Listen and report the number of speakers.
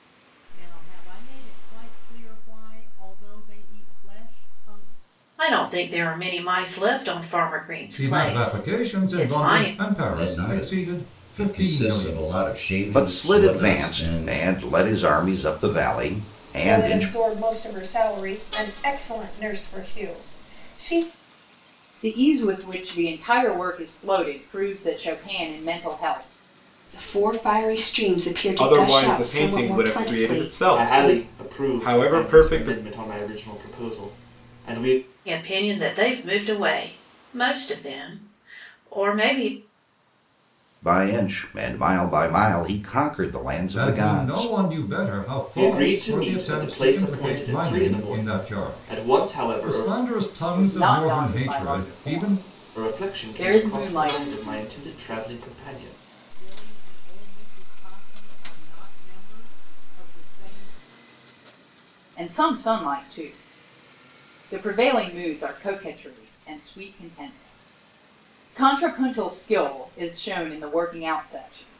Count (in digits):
10